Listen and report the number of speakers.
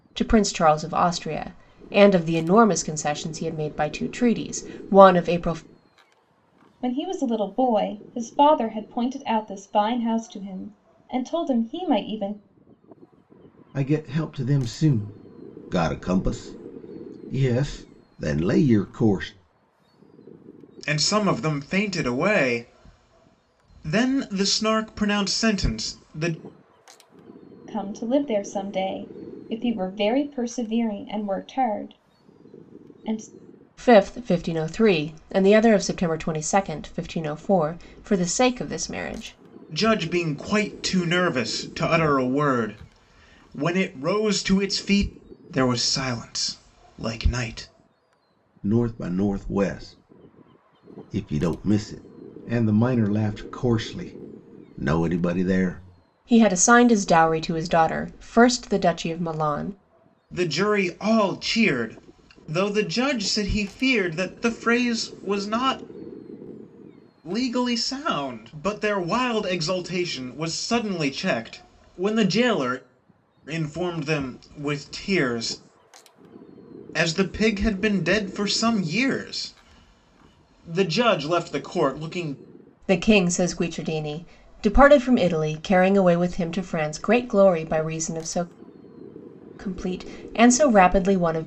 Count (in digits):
4